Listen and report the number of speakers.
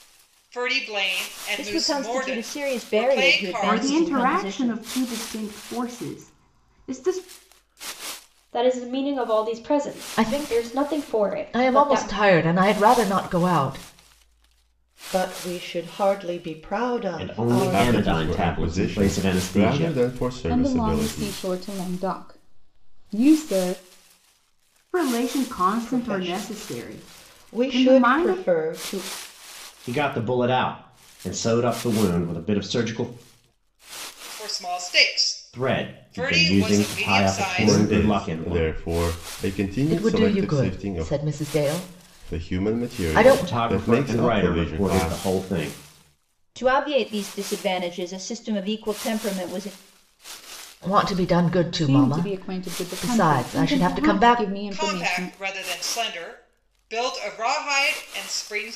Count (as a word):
nine